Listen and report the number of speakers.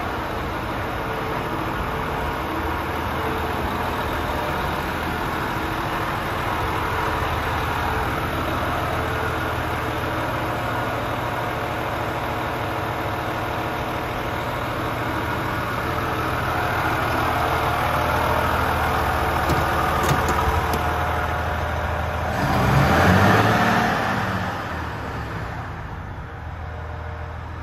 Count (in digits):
0